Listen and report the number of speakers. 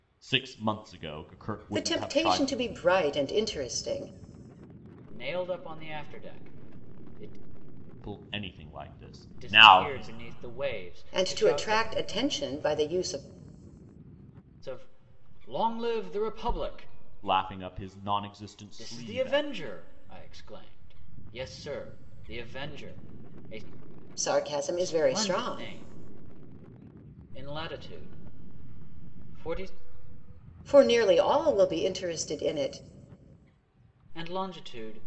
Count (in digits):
3